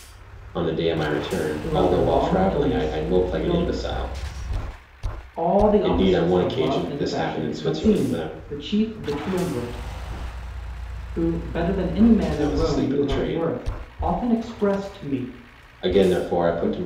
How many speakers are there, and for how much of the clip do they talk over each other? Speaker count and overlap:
two, about 34%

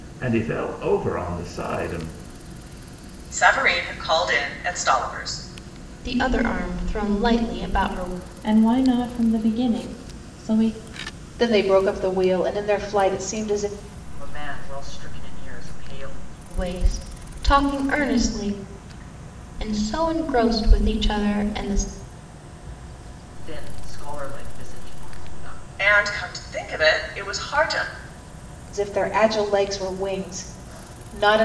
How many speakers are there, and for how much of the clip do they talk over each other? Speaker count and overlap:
six, no overlap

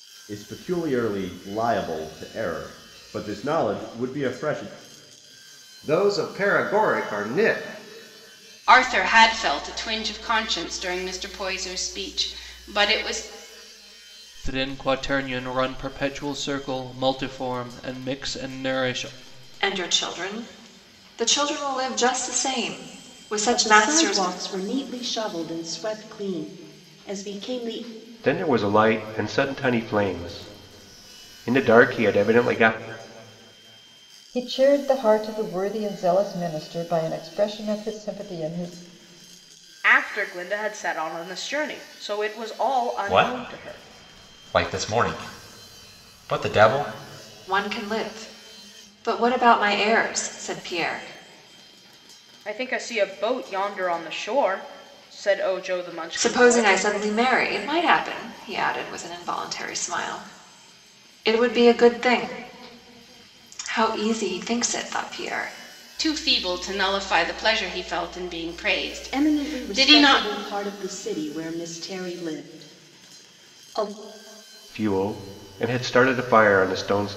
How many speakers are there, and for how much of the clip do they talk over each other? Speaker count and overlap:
ten, about 4%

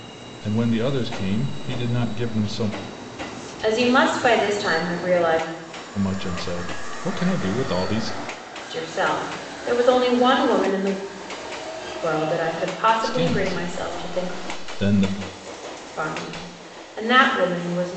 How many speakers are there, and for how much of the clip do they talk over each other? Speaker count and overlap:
two, about 8%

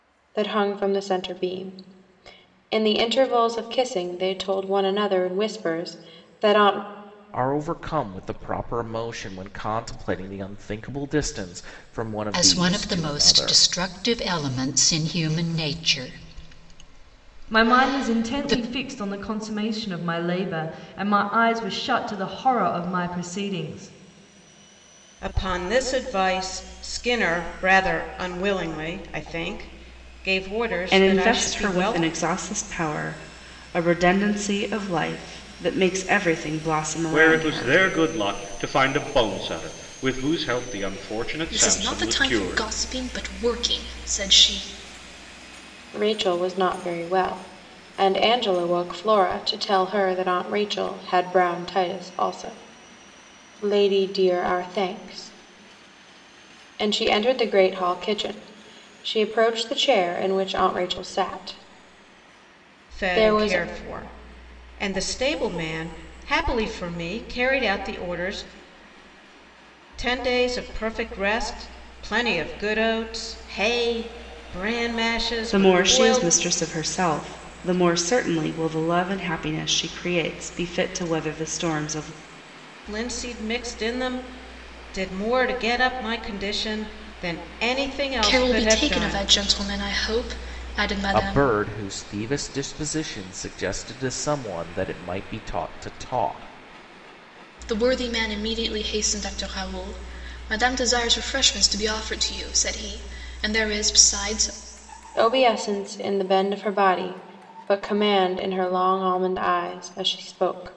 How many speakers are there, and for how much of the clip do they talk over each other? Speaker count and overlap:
eight, about 8%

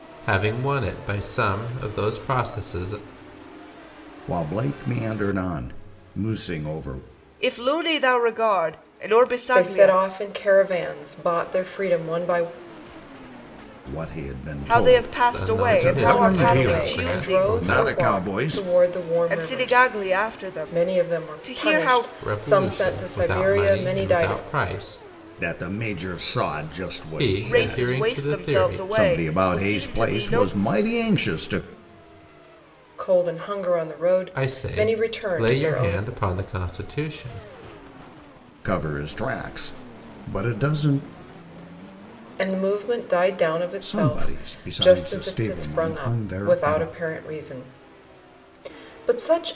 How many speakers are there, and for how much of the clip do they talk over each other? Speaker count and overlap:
four, about 36%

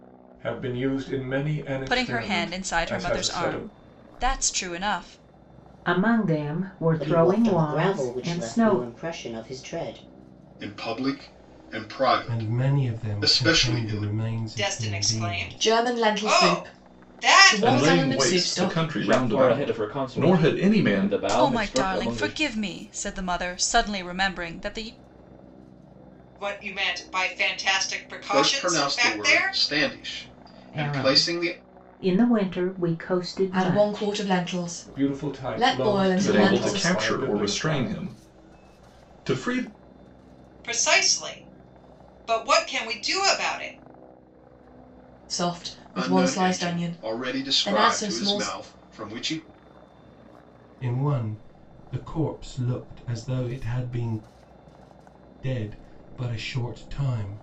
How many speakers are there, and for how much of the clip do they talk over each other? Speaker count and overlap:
ten, about 38%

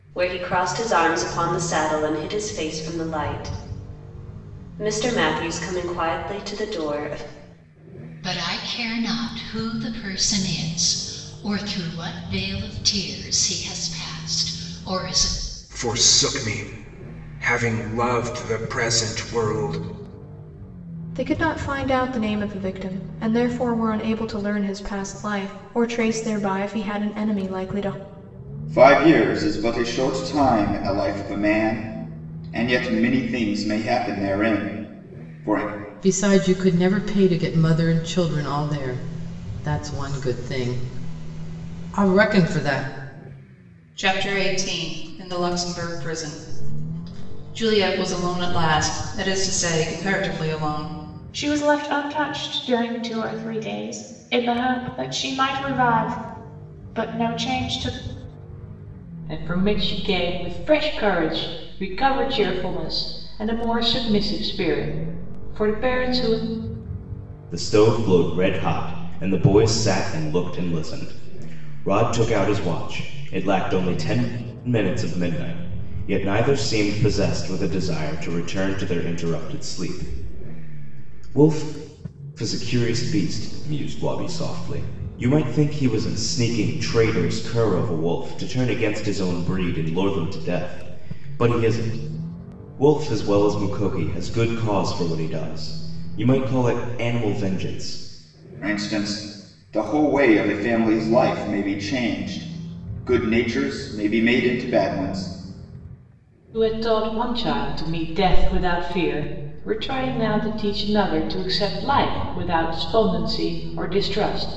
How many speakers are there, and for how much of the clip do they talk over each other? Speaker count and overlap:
ten, no overlap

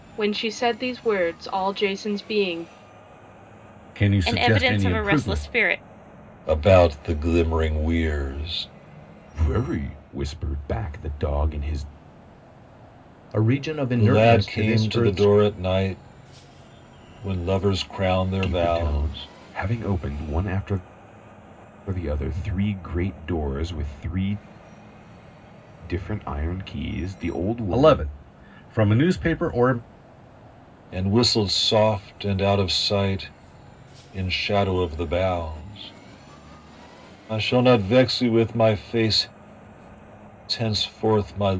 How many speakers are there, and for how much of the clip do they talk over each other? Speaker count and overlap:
six, about 10%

